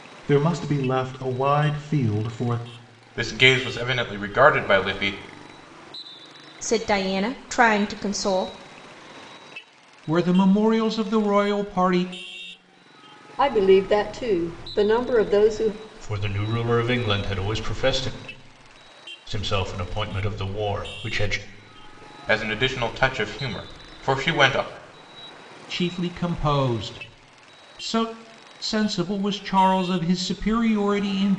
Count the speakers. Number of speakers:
6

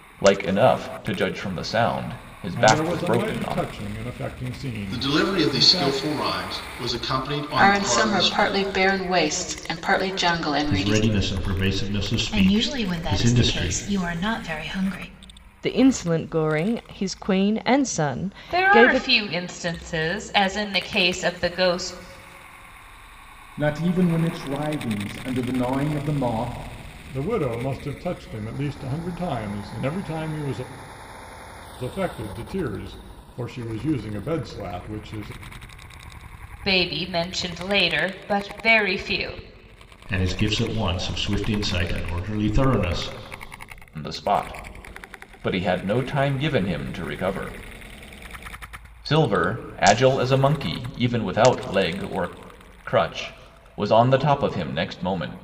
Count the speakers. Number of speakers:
9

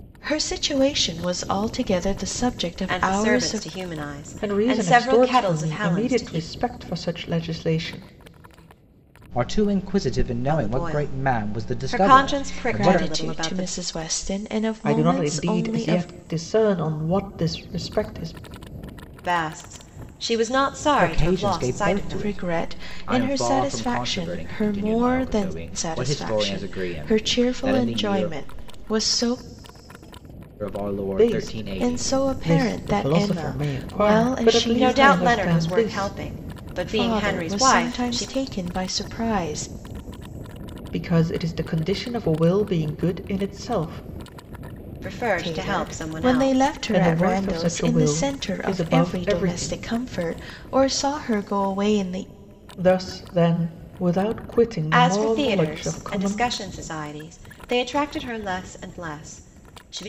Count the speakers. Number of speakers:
4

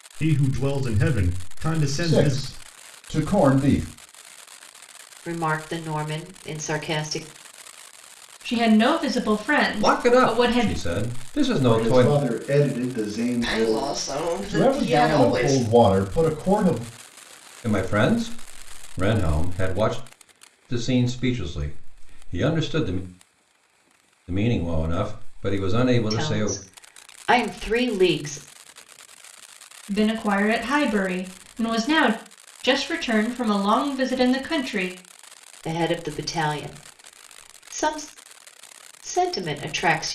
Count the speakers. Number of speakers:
7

